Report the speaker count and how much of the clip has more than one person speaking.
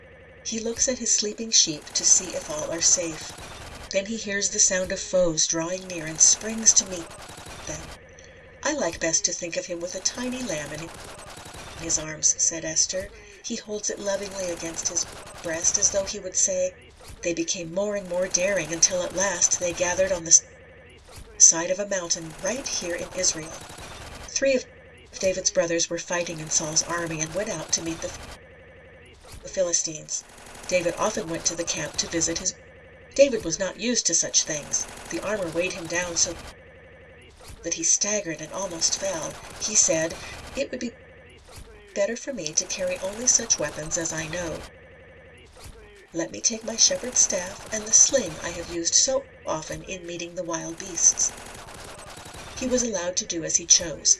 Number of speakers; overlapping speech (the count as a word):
one, no overlap